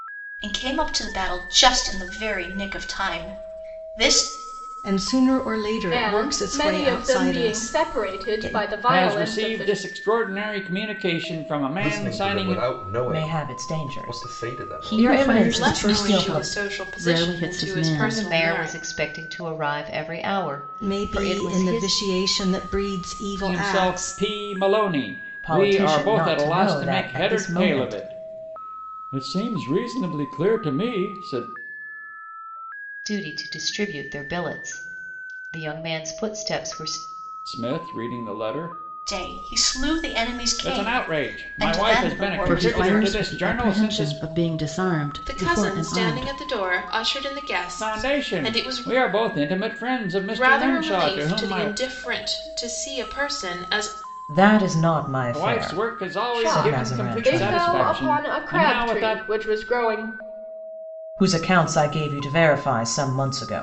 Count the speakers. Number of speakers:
nine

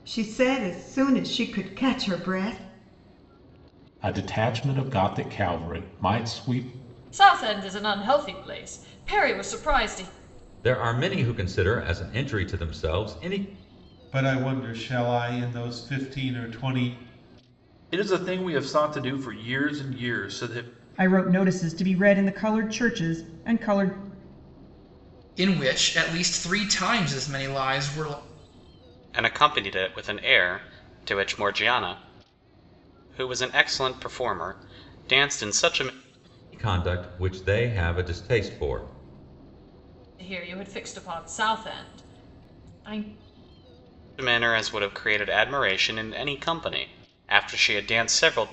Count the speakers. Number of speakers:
nine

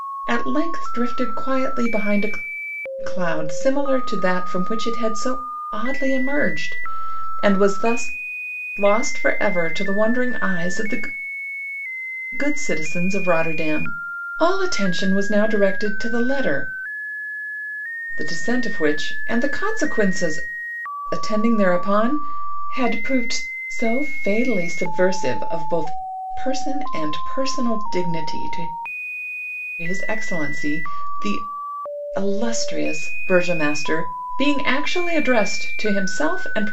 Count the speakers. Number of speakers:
one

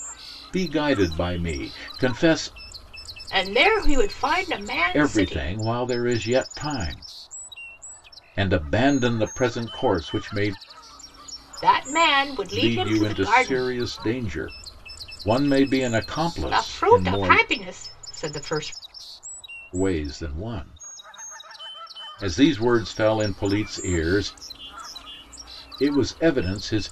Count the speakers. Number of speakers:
two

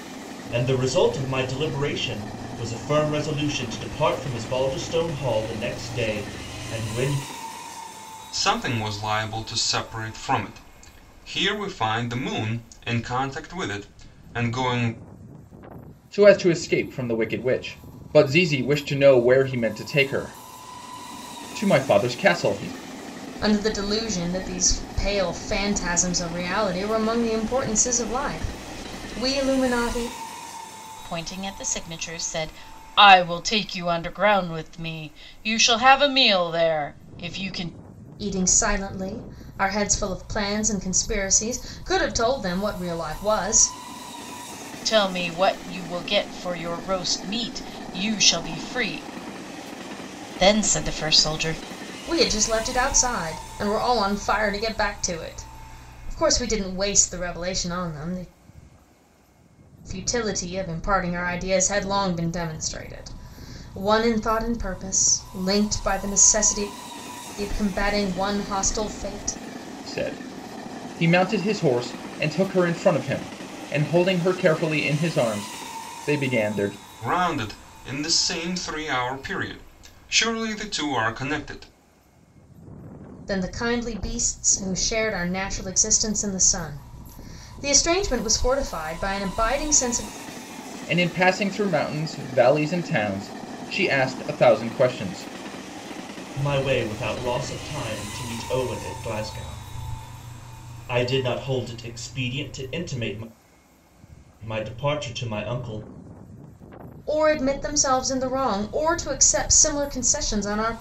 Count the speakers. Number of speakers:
five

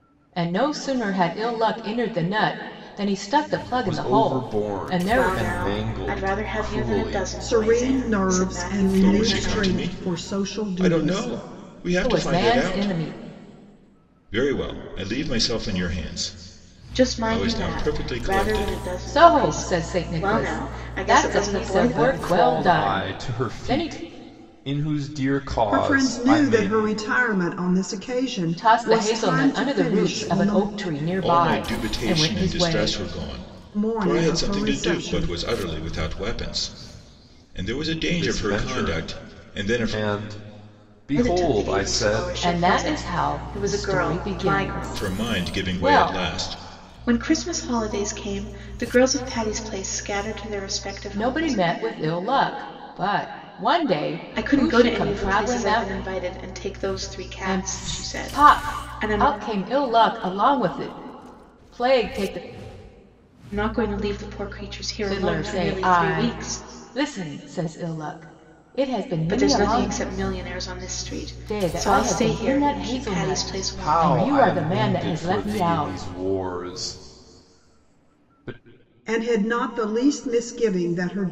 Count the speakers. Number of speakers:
five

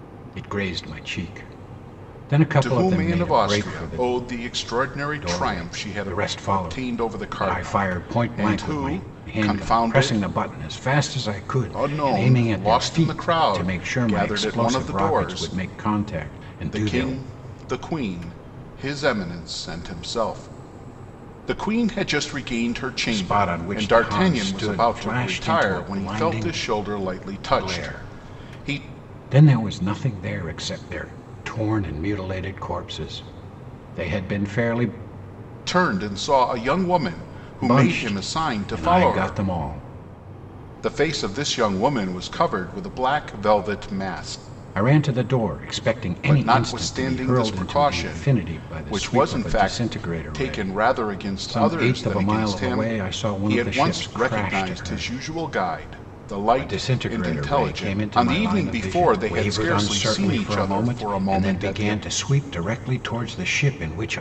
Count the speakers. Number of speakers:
two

